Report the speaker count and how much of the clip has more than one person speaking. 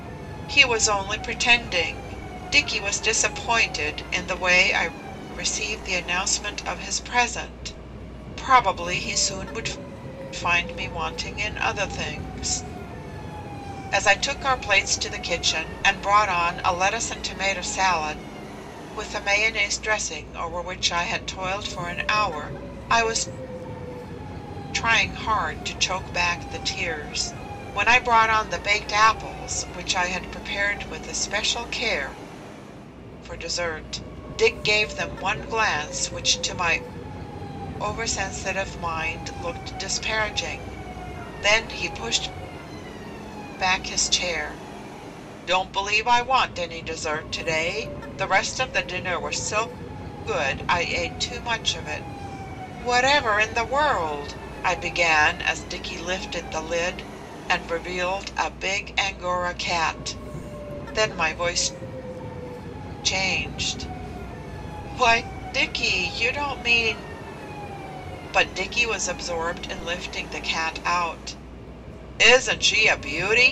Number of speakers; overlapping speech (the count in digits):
1, no overlap